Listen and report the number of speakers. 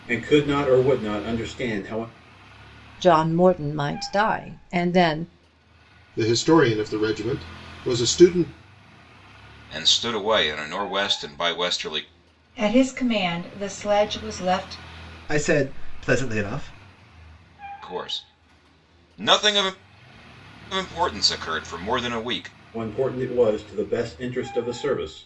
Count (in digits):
6